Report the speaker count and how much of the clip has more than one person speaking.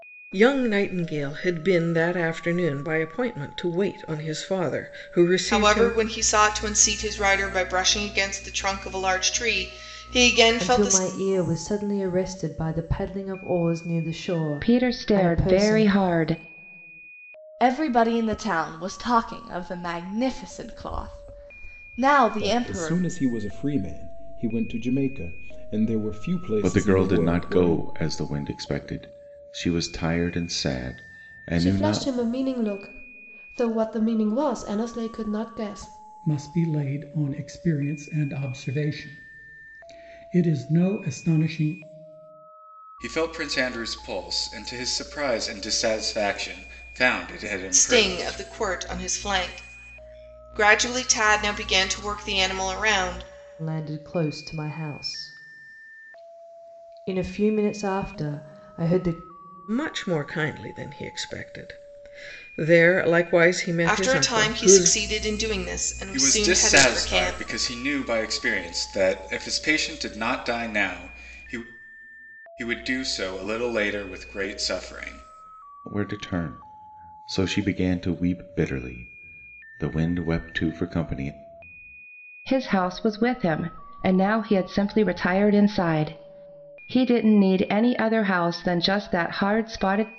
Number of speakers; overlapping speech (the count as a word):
ten, about 9%